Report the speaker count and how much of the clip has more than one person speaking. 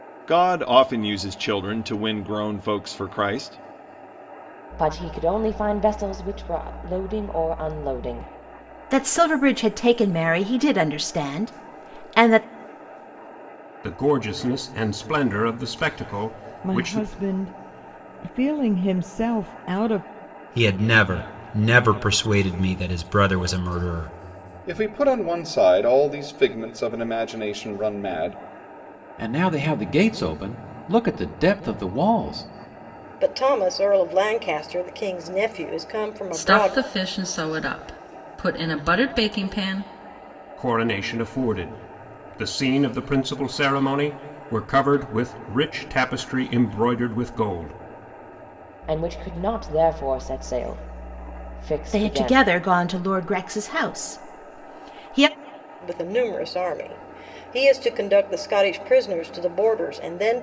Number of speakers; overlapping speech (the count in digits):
10, about 3%